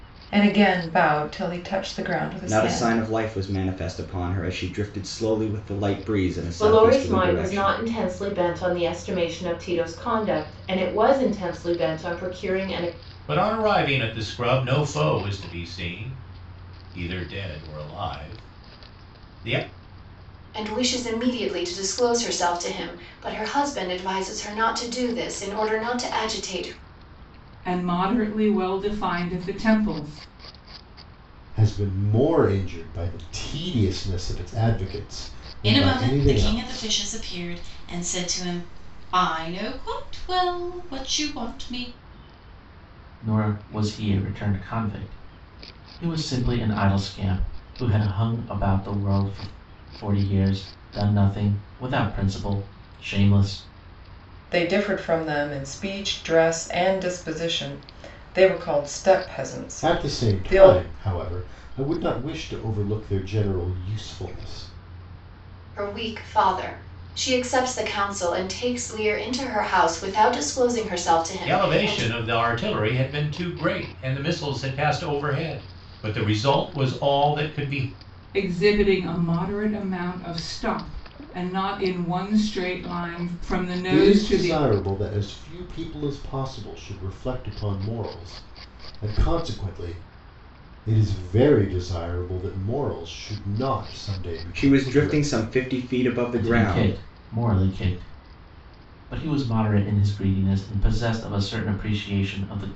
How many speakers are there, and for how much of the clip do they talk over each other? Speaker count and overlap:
9, about 7%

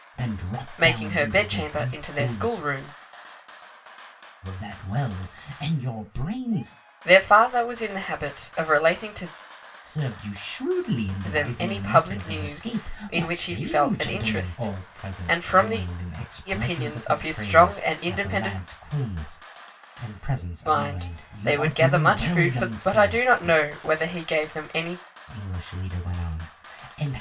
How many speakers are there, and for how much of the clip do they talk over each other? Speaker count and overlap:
2, about 43%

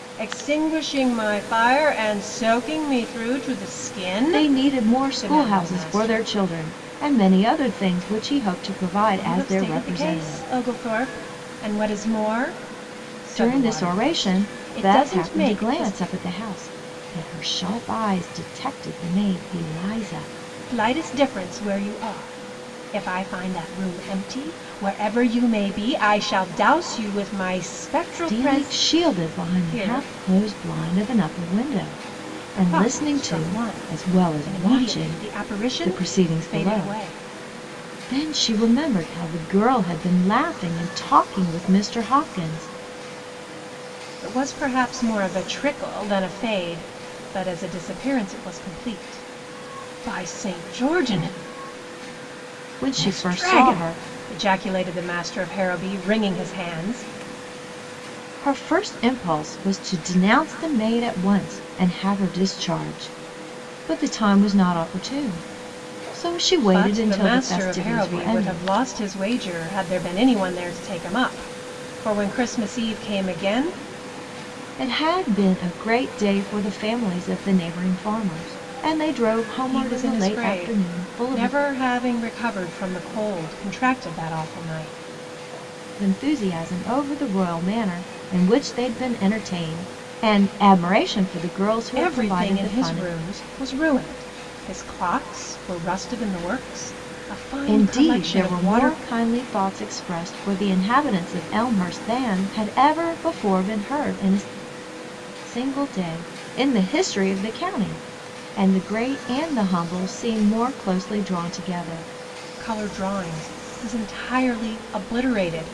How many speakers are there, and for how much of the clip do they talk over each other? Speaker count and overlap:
2, about 17%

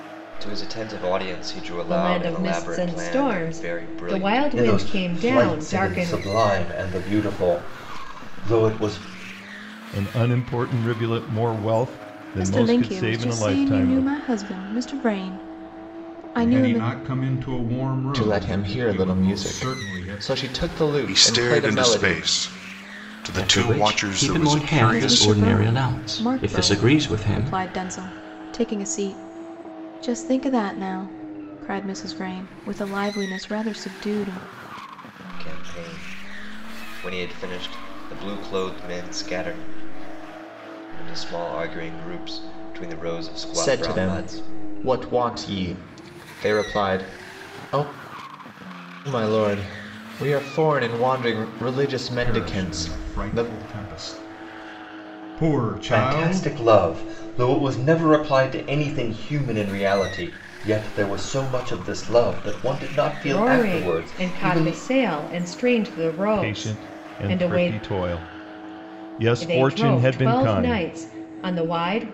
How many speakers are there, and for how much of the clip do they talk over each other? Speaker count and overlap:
9, about 30%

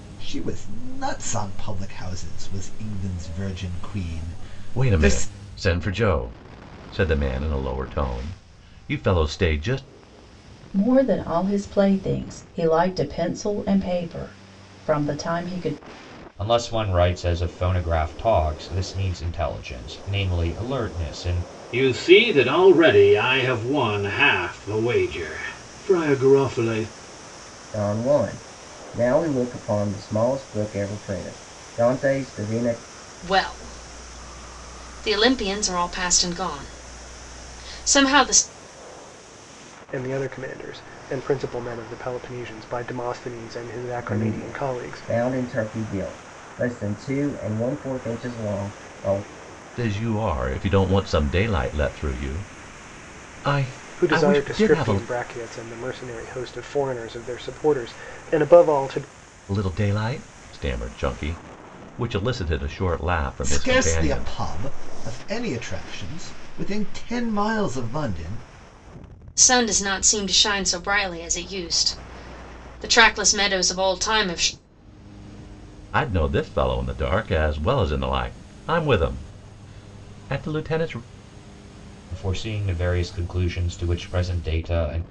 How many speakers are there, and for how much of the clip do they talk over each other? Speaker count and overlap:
8, about 4%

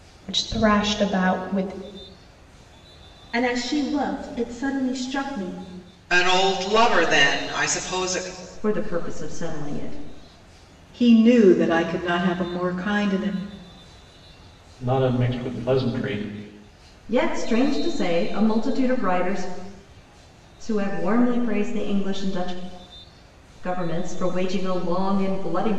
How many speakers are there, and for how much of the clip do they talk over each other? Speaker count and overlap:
6, no overlap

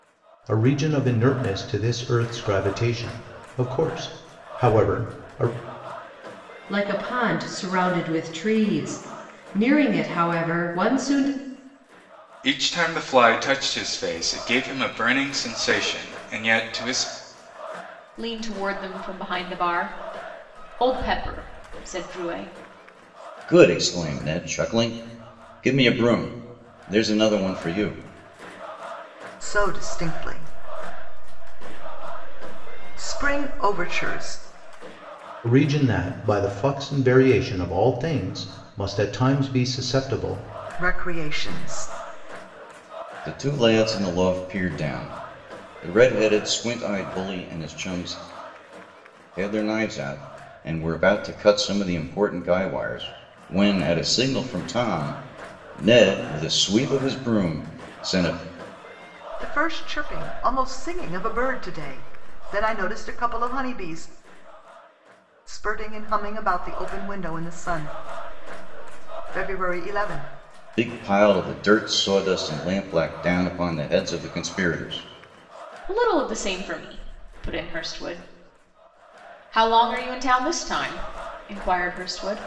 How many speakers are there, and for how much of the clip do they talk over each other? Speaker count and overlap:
6, no overlap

